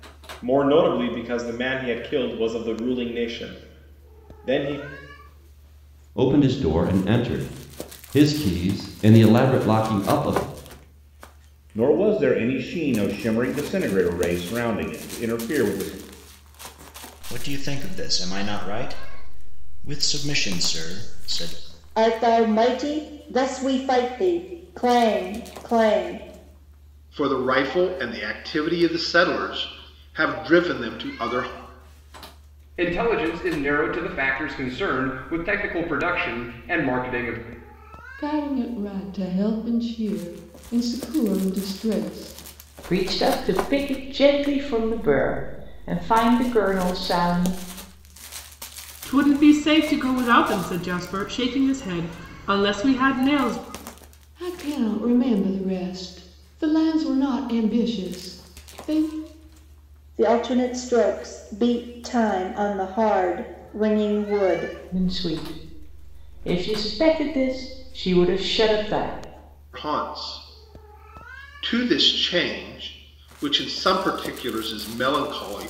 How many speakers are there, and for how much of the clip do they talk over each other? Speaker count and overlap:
10, no overlap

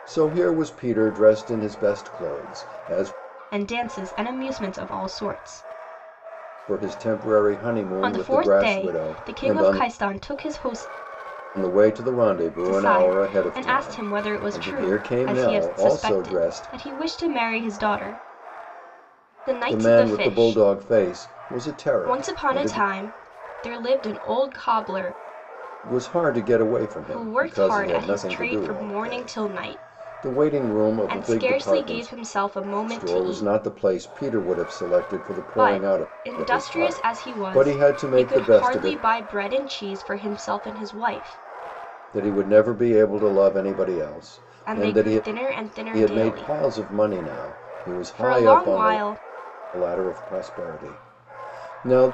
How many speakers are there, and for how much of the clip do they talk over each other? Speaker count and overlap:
2, about 34%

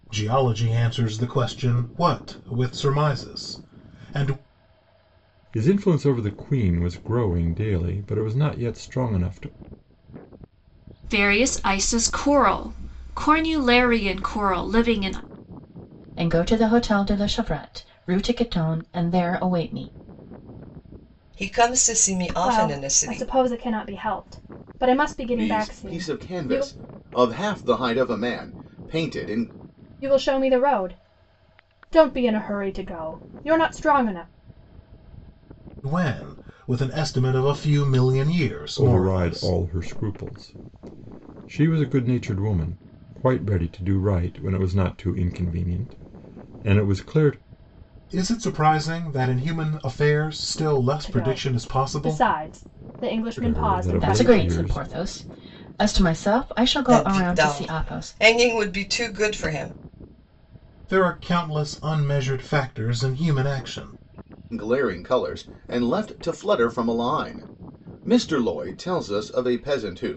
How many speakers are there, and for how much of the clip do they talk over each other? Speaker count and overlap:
7, about 10%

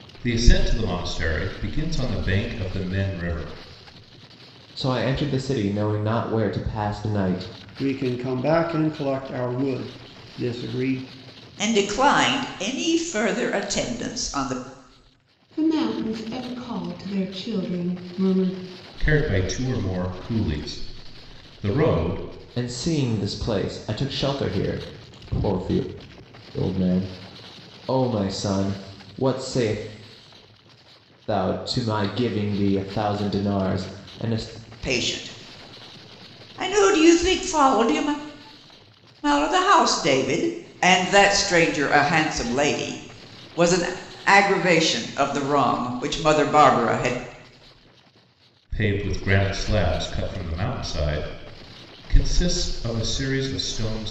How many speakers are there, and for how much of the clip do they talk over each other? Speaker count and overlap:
5, no overlap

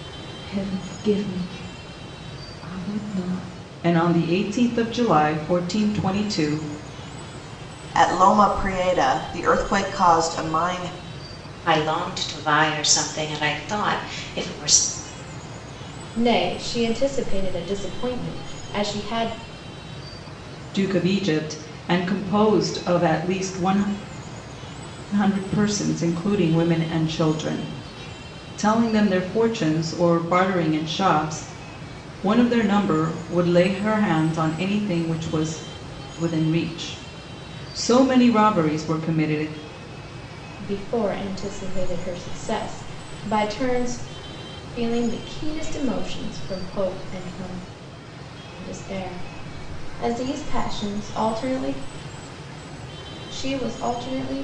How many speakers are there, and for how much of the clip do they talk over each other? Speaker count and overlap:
5, no overlap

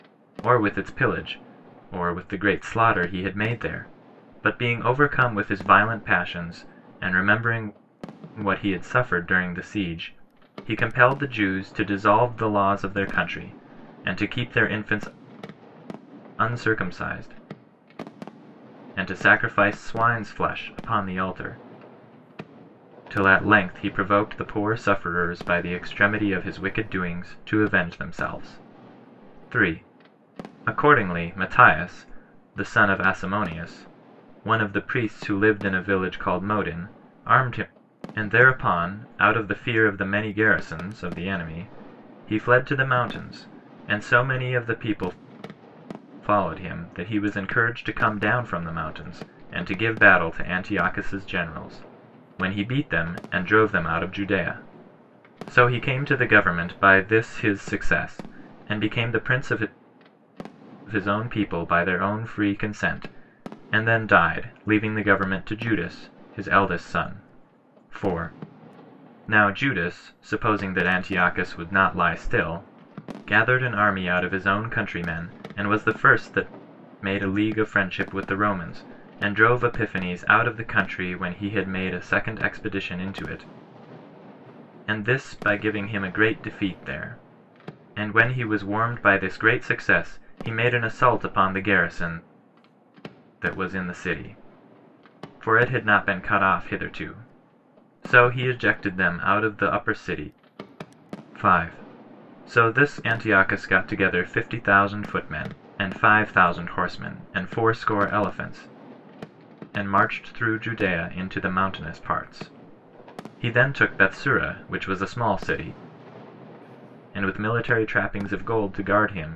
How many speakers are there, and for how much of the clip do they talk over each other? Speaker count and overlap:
1, no overlap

